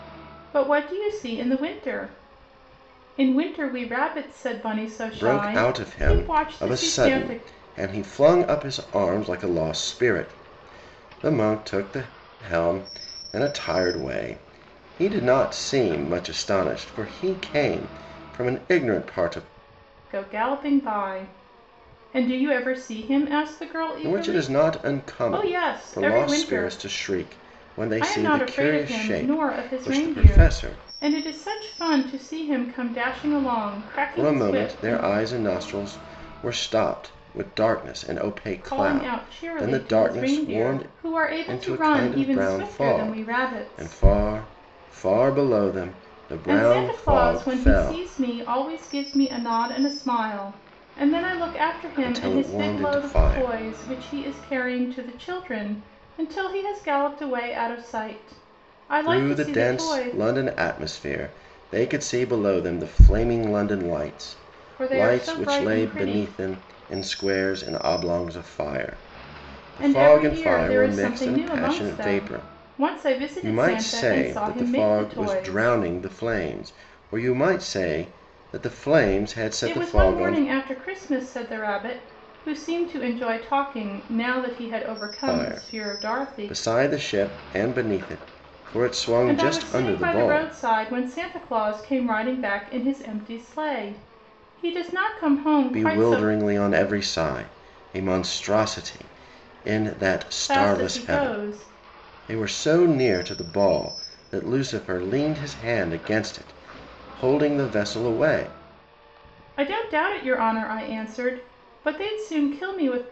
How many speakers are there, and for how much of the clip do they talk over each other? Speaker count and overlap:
two, about 27%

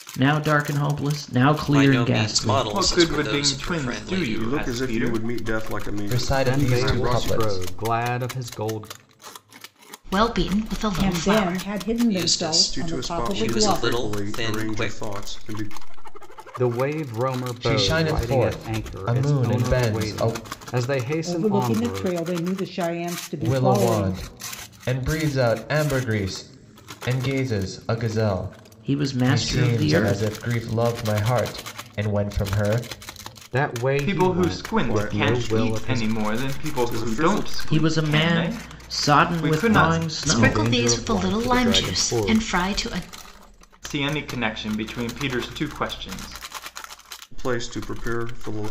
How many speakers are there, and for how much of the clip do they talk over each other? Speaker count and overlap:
eight, about 48%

